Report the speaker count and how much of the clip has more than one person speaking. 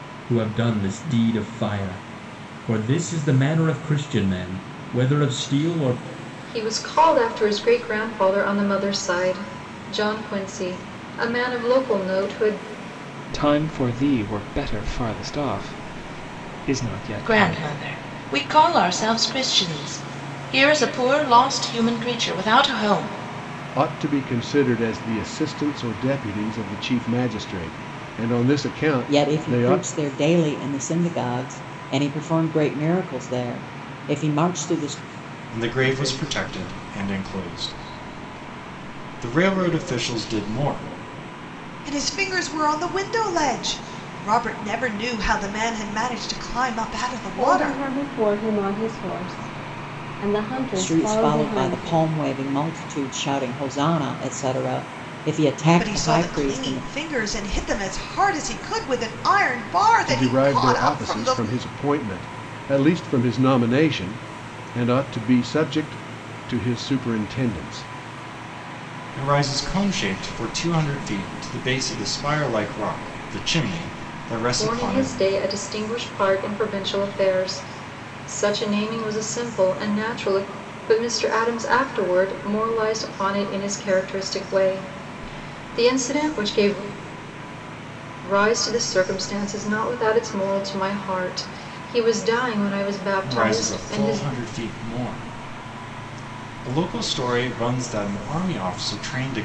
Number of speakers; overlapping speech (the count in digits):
9, about 8%